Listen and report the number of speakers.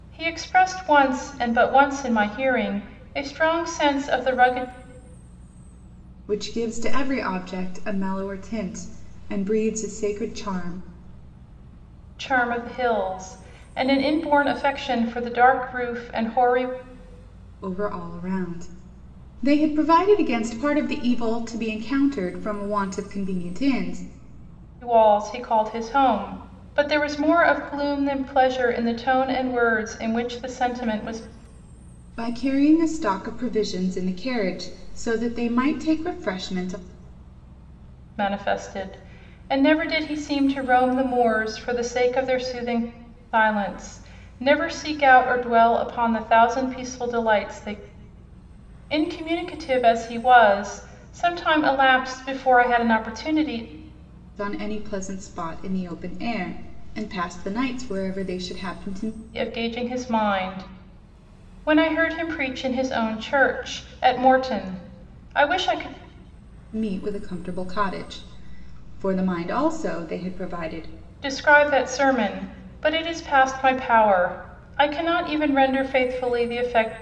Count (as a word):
two